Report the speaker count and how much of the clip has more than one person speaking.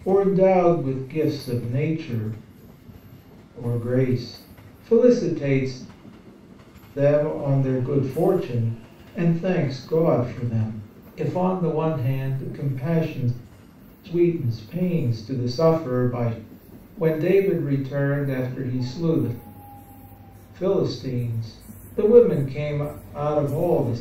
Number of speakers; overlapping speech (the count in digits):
1, no overlap